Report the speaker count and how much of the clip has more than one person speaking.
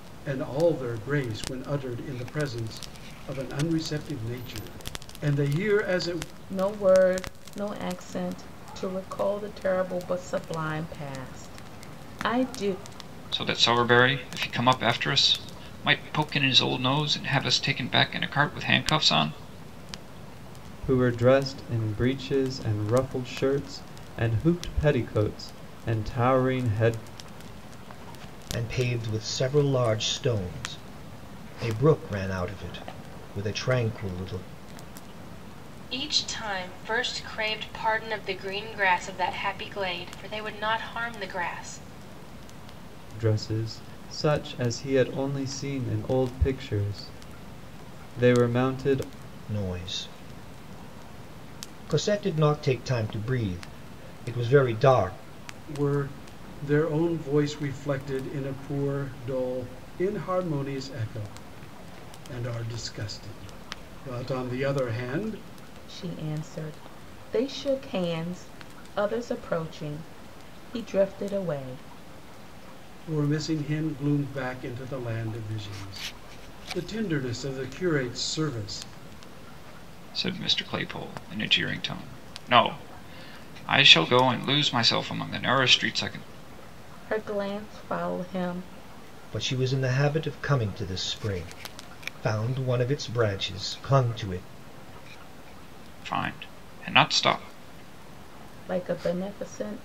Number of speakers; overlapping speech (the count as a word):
six, no overlap